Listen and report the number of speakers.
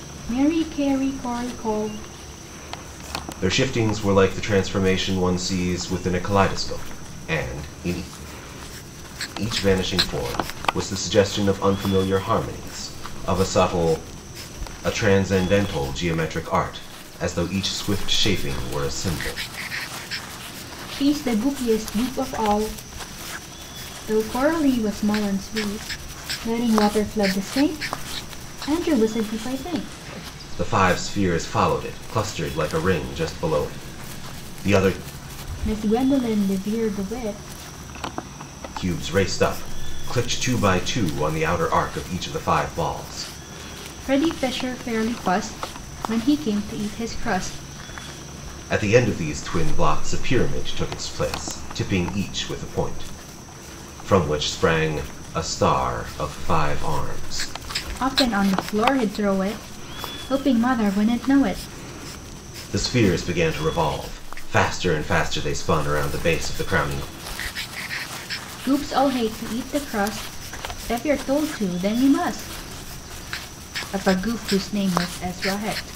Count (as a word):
two